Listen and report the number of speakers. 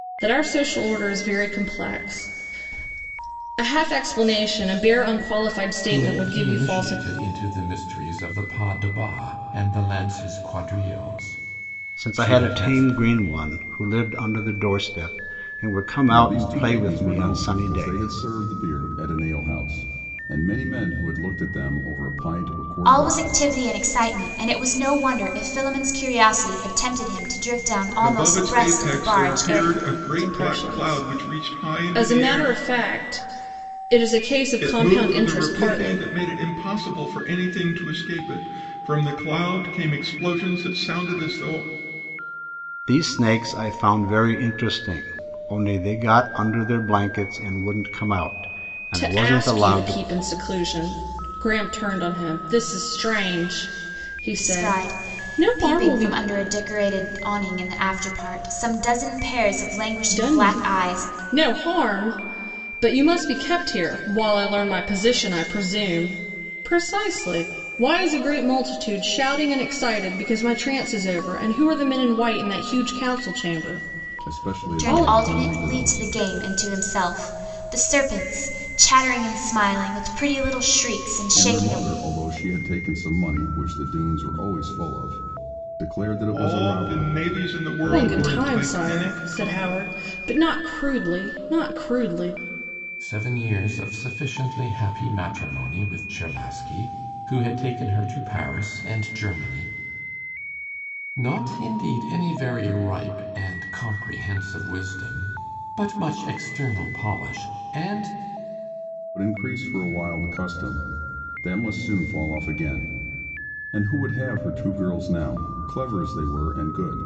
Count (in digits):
6